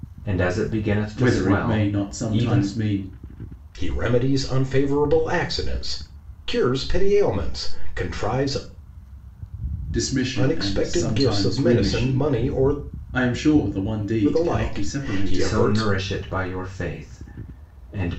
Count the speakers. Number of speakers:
3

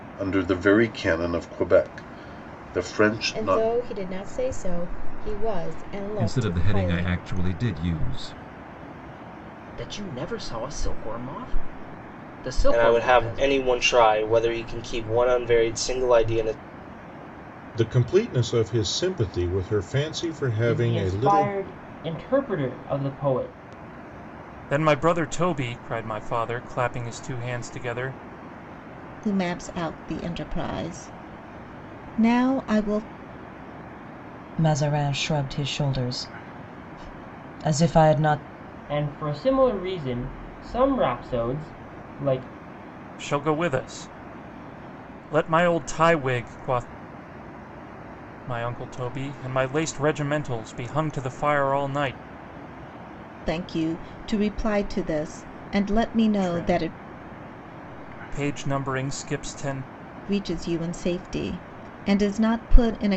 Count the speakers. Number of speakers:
10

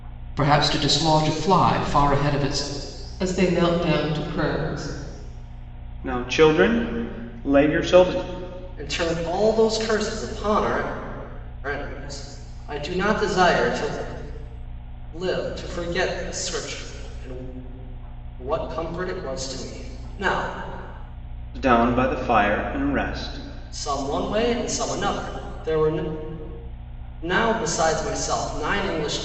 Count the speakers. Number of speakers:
4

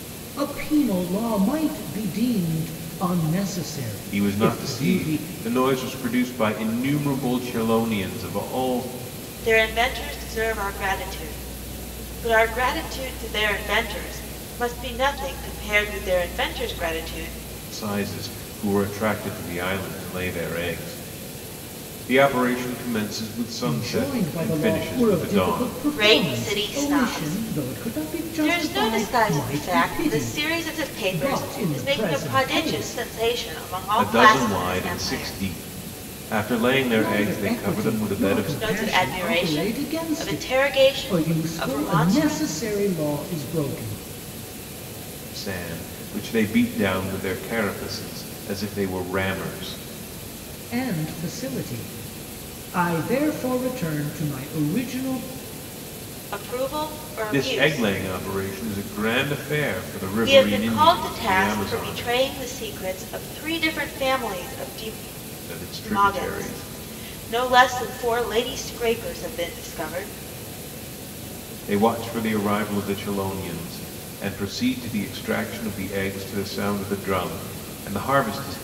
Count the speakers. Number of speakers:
3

